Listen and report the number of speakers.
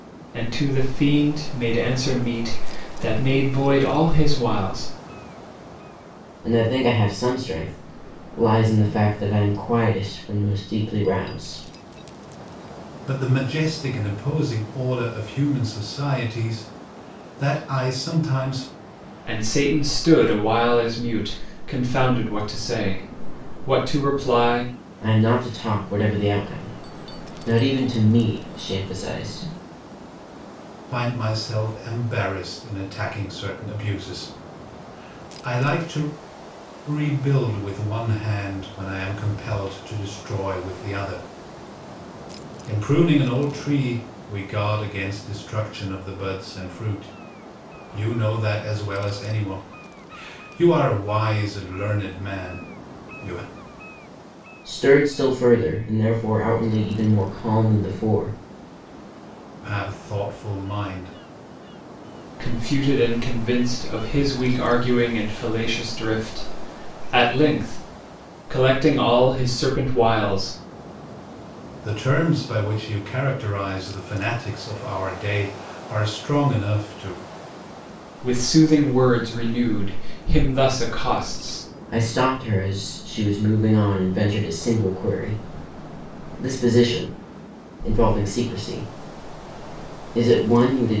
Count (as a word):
three